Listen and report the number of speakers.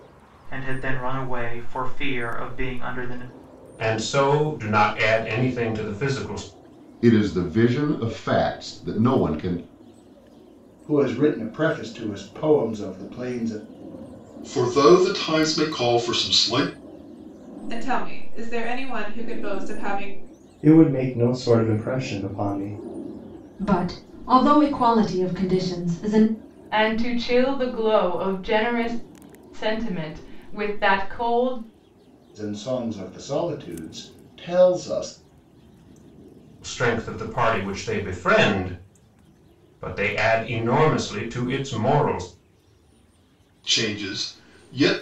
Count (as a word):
nine